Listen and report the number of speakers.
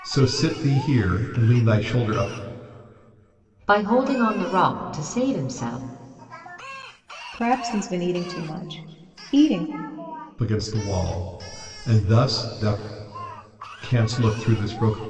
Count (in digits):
3